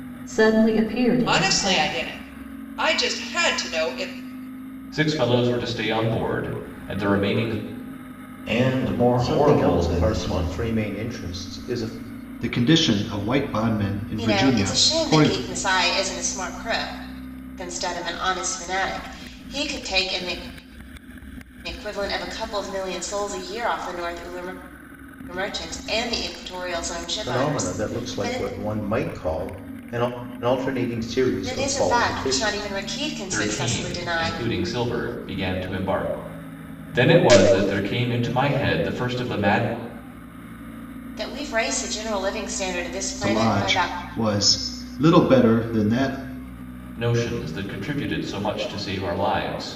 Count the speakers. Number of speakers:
7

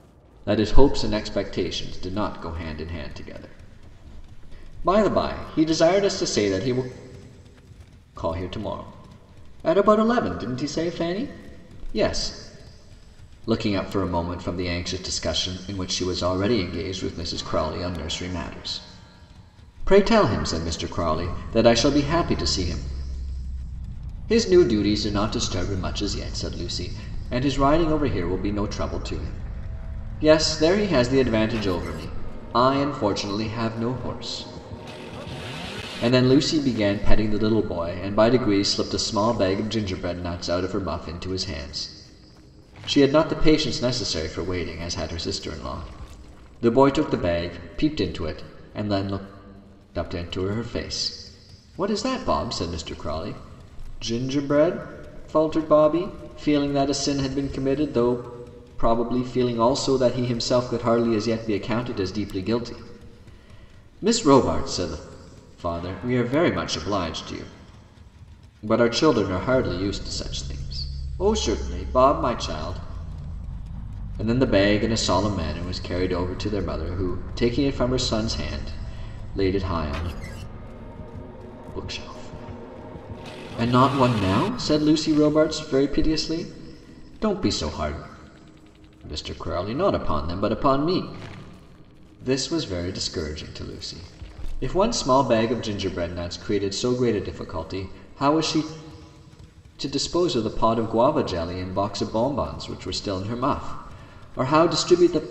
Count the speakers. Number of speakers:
1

